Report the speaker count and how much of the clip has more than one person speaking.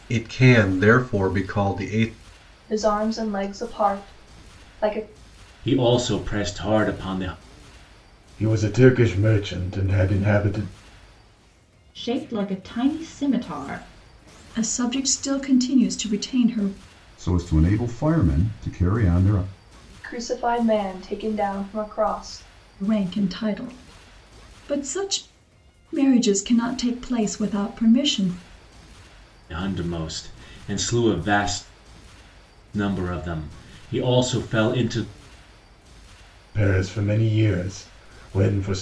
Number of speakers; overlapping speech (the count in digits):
7, no overlap